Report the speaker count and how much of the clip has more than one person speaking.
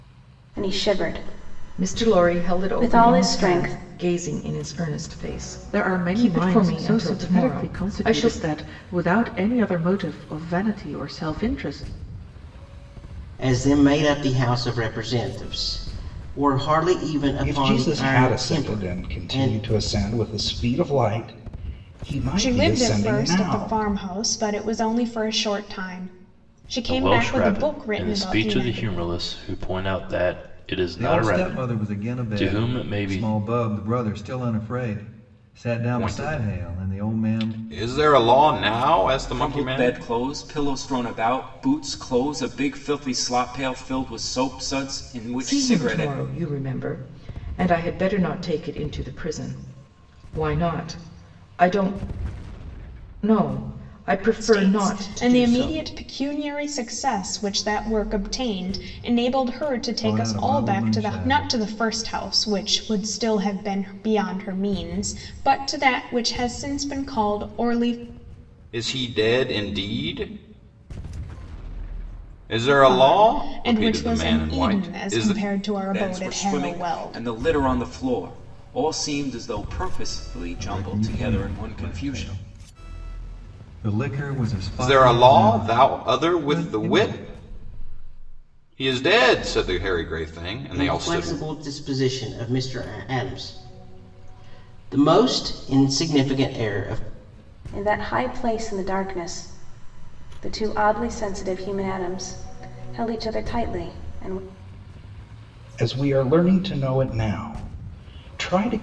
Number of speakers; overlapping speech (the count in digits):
10, about 25%